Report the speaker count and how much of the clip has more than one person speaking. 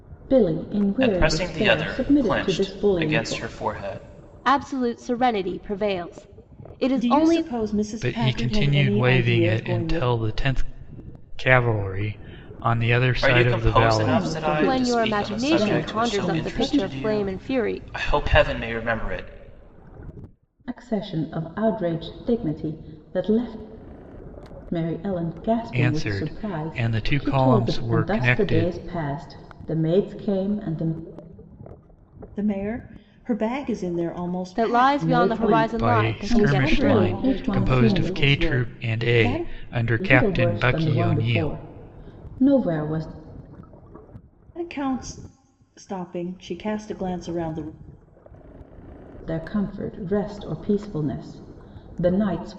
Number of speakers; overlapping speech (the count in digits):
5, about 37%